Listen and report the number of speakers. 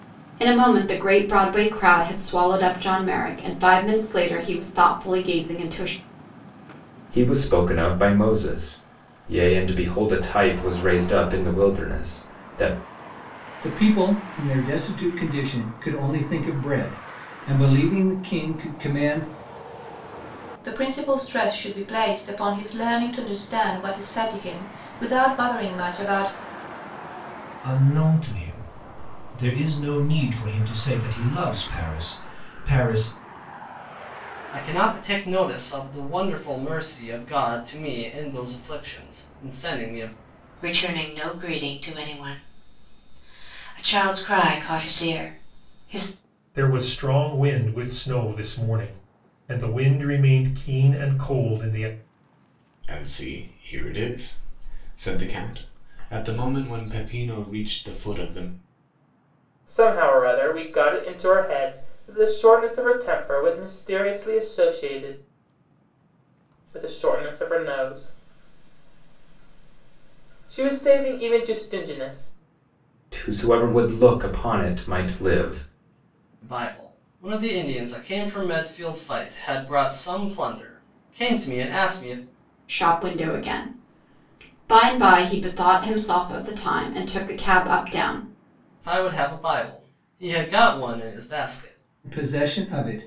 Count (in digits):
10